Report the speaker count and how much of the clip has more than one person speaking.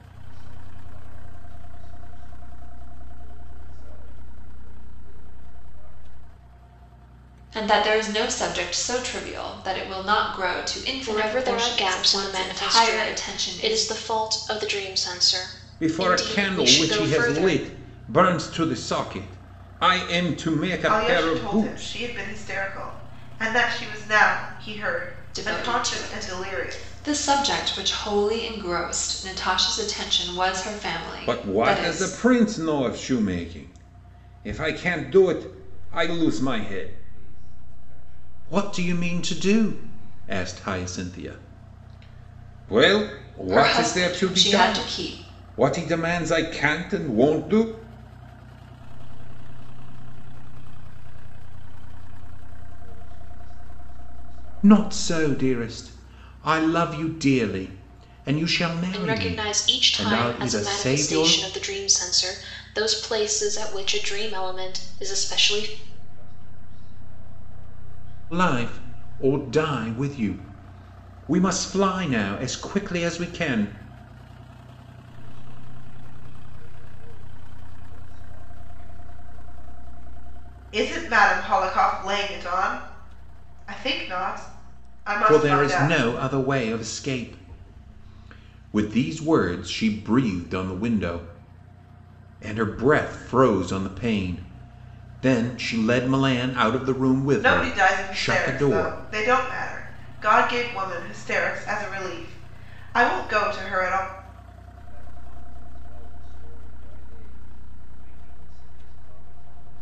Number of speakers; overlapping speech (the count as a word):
five, about 21%